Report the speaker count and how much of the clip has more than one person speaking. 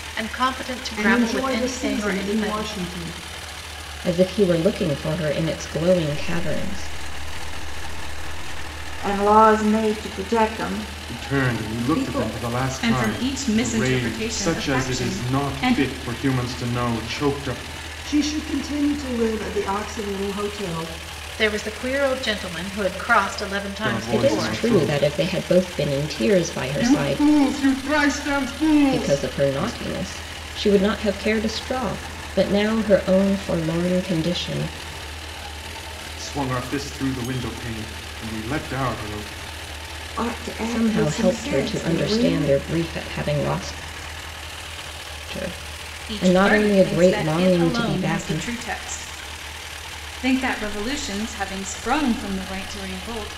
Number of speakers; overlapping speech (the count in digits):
7, about 26%